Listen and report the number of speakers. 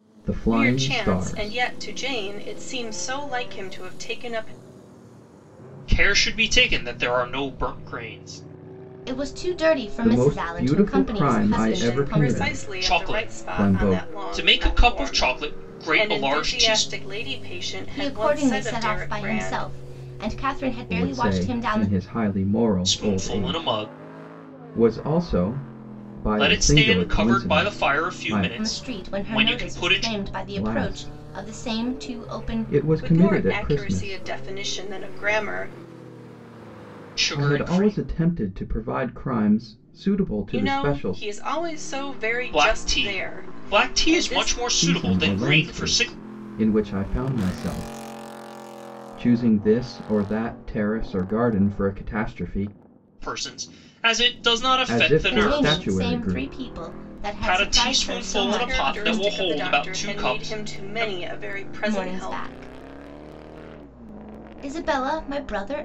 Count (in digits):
4